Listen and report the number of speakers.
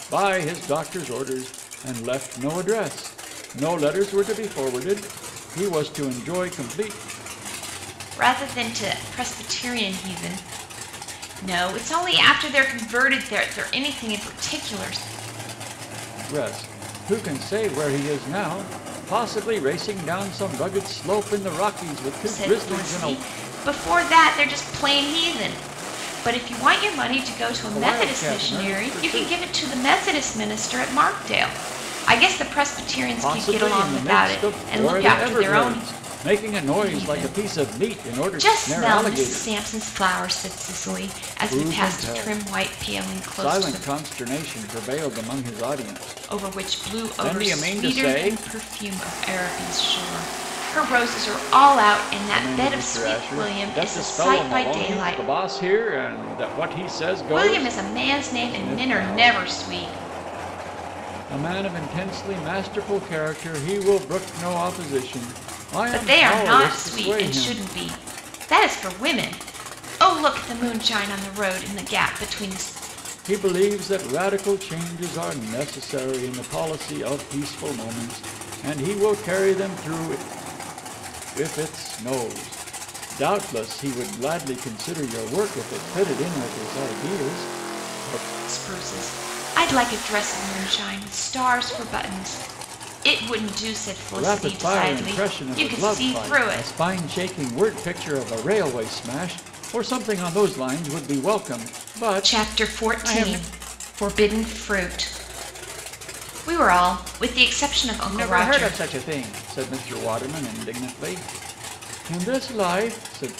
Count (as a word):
two